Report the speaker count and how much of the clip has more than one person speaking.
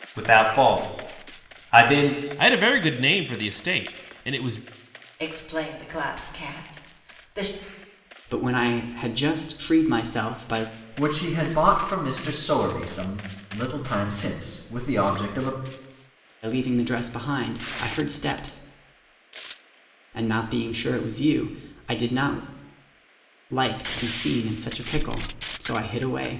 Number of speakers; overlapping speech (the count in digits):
5, no overlap